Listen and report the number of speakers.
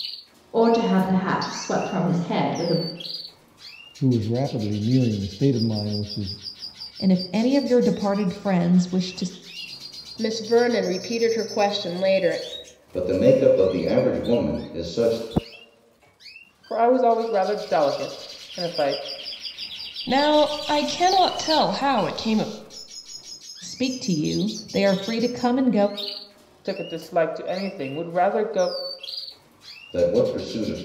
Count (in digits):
7